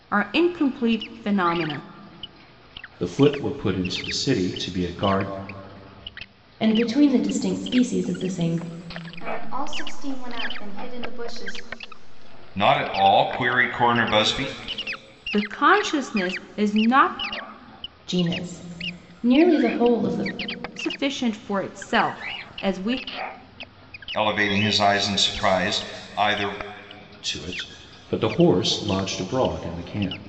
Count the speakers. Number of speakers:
five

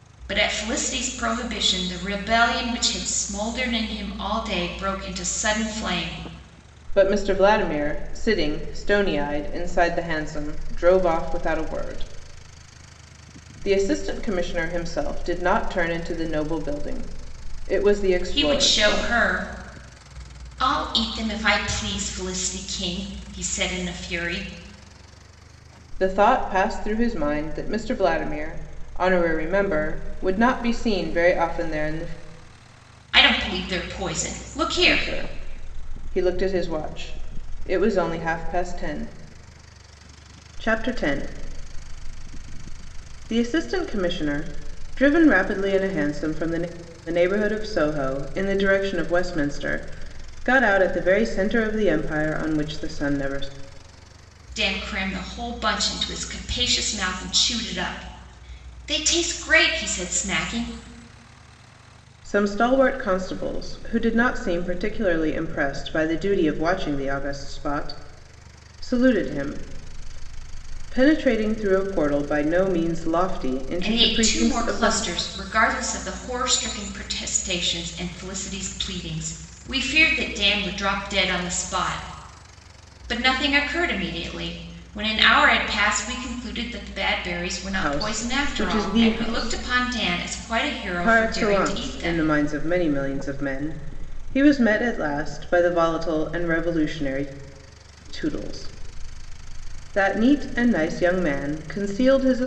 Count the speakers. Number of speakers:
two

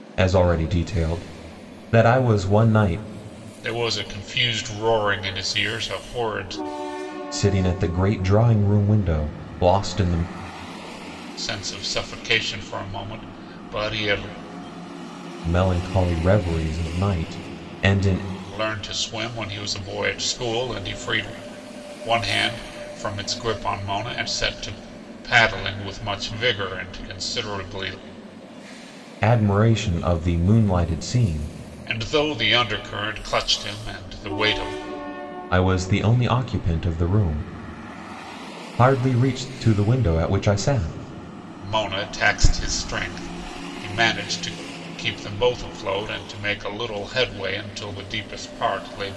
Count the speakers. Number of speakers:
two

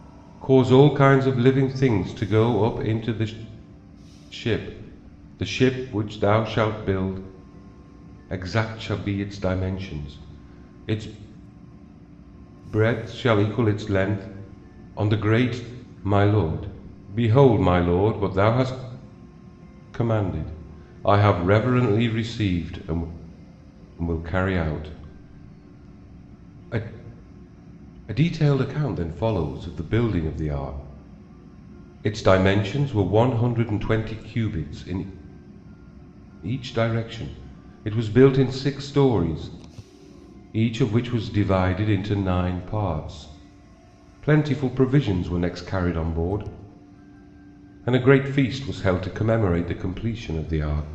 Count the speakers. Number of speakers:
one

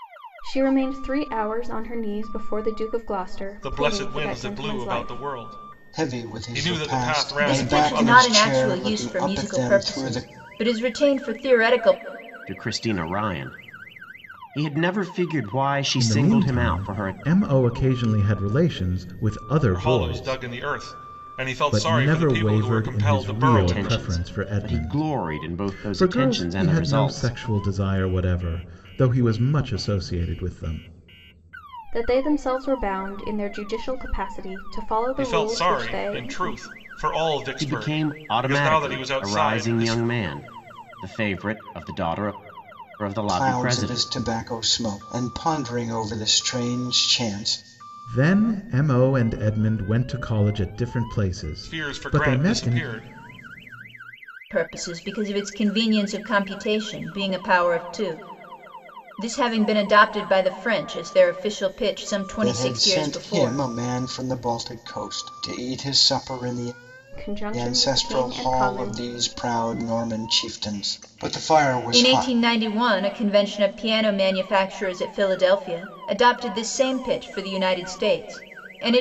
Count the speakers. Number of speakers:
six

